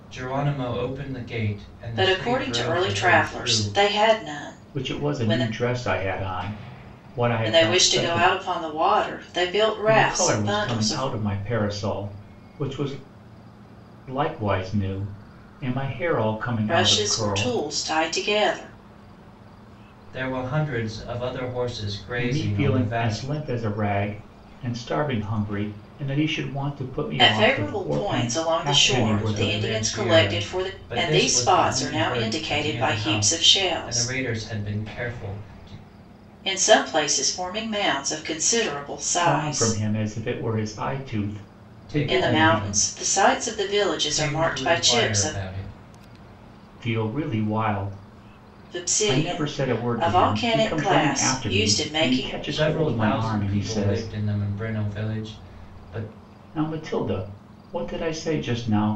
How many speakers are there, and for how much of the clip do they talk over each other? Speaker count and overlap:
three, about 37%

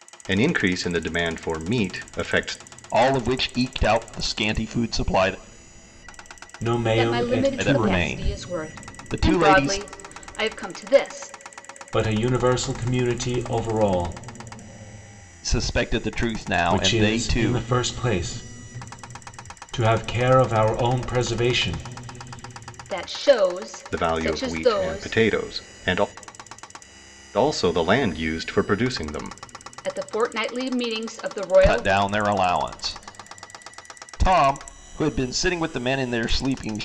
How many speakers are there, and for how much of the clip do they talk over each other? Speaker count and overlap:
four, about 15%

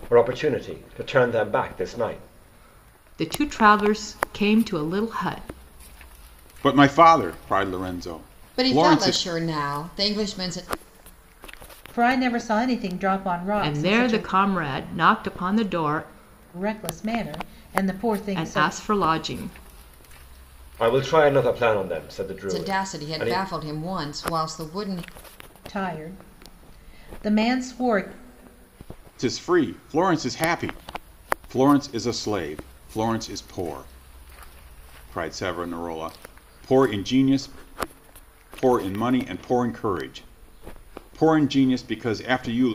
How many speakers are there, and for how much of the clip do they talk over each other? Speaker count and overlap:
five, about 6%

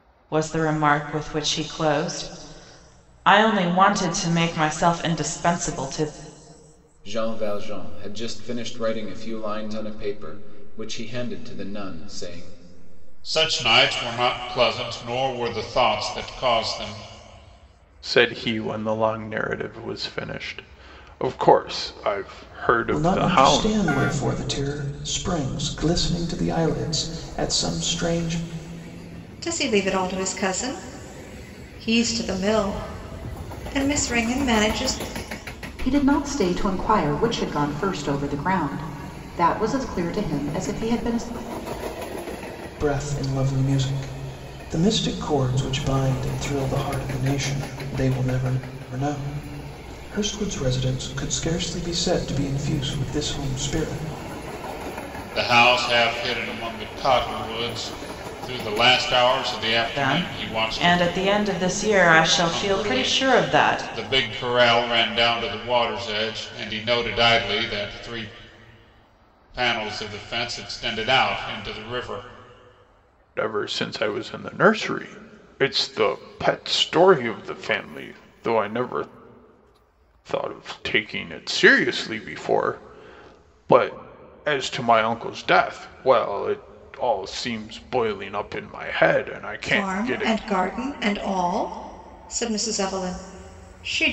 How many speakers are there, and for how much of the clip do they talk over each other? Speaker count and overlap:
seven, about 5%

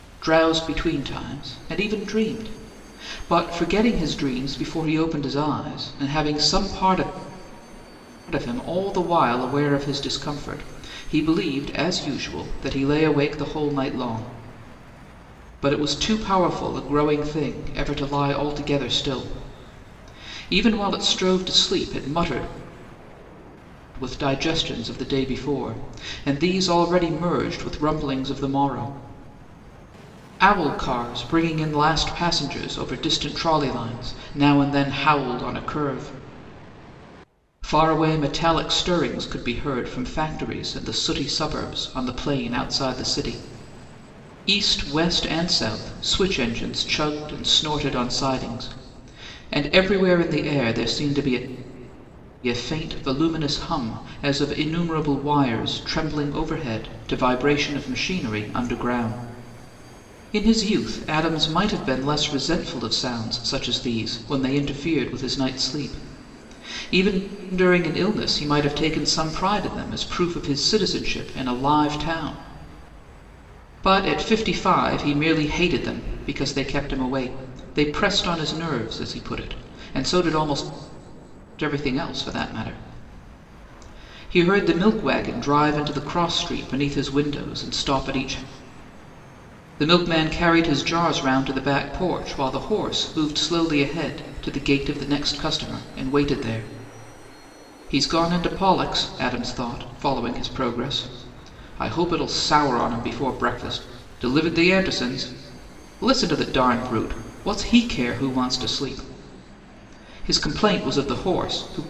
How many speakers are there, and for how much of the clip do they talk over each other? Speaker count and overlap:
one, no overlap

